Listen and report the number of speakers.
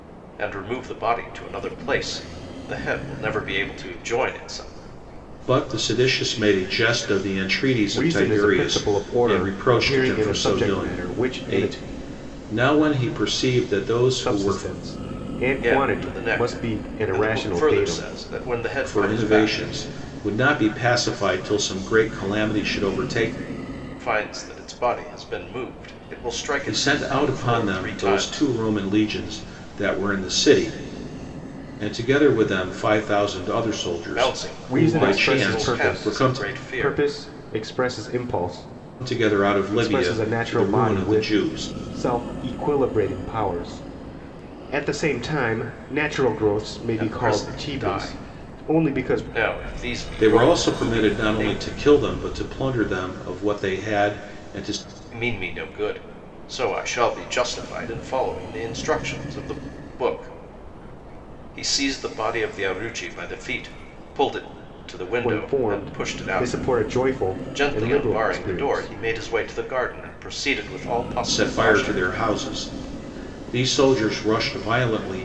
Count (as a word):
three